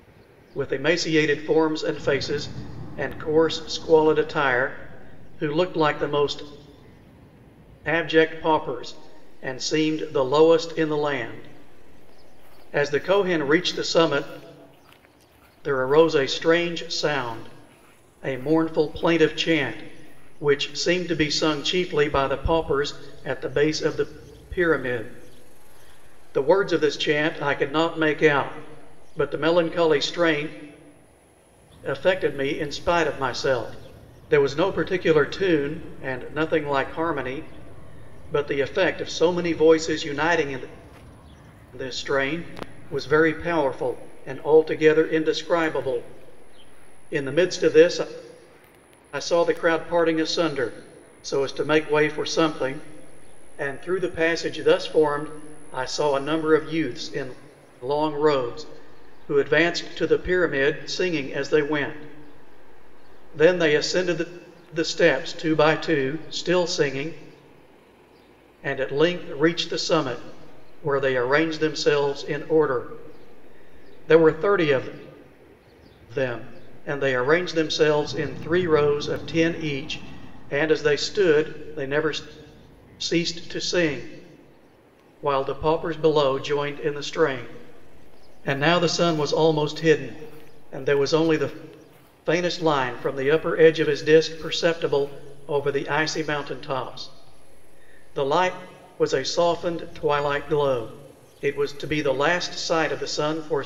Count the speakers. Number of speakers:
1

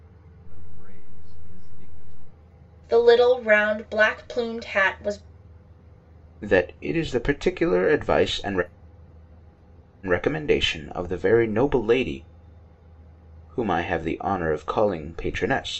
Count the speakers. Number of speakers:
3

